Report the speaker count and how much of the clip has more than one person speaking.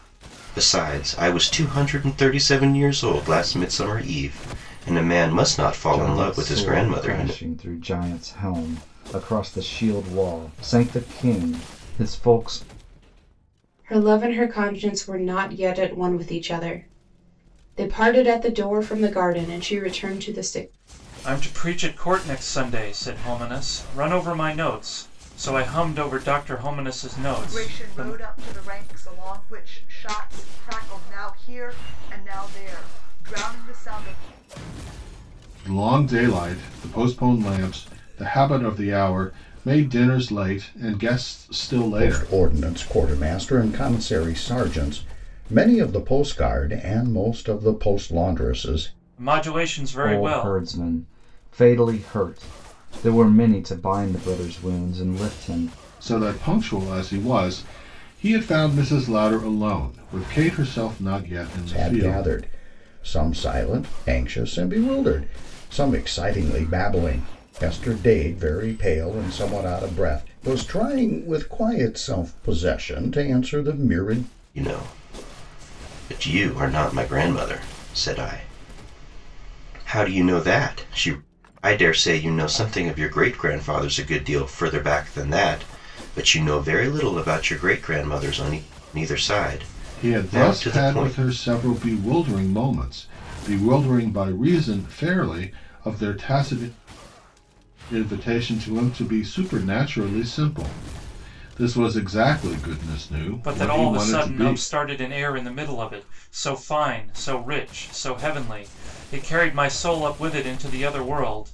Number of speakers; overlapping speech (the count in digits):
7, about 6%